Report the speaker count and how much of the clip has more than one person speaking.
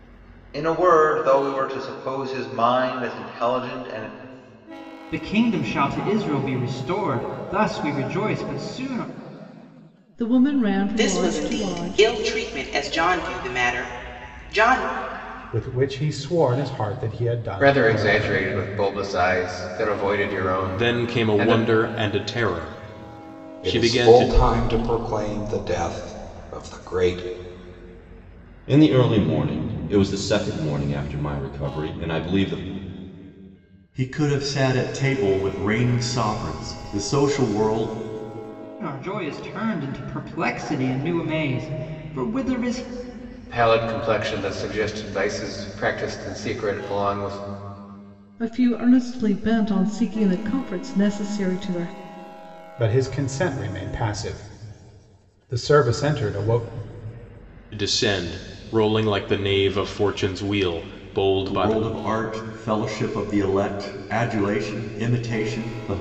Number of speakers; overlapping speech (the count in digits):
10, about 6%